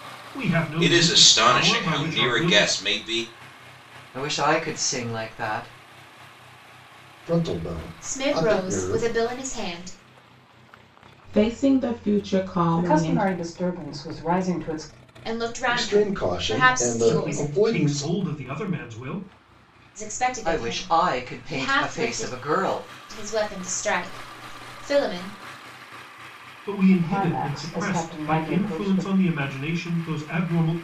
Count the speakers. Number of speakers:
7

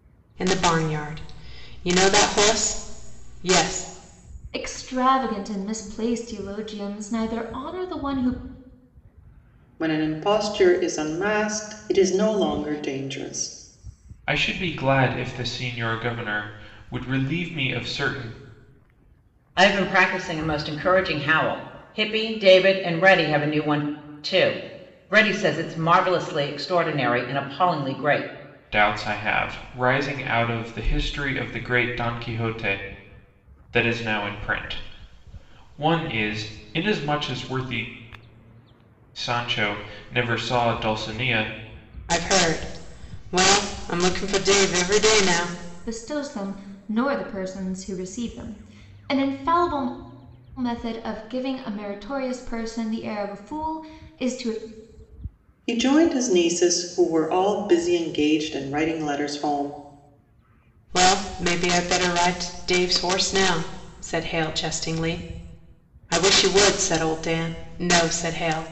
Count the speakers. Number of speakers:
5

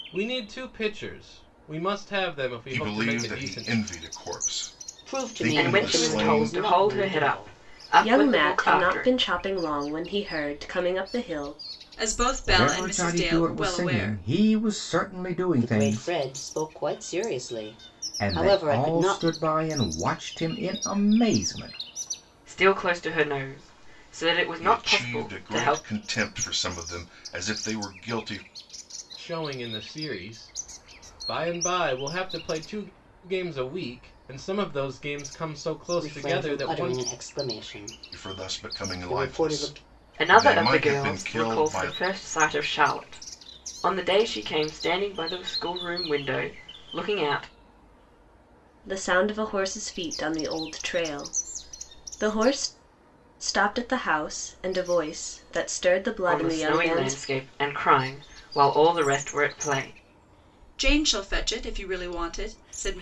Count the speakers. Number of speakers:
7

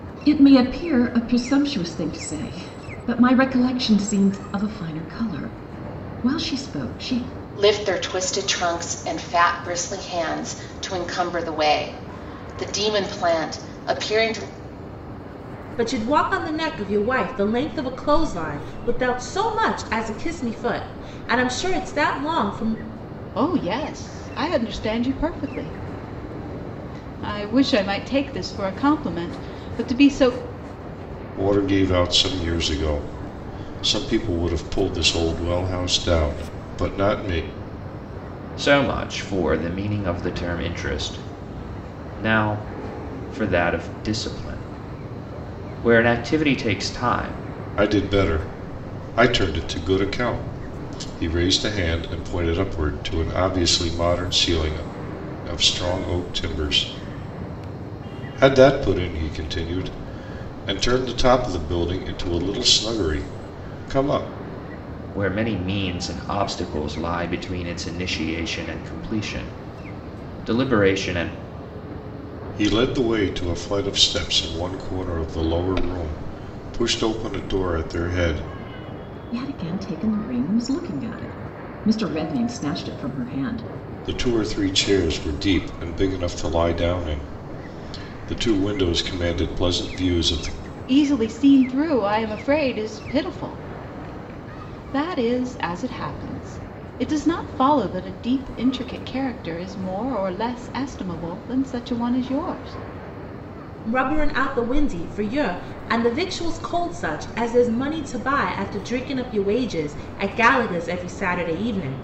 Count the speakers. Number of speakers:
6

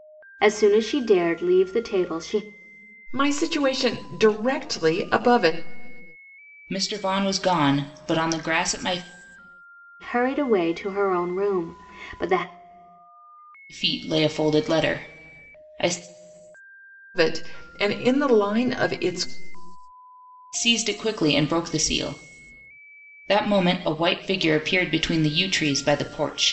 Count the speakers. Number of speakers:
3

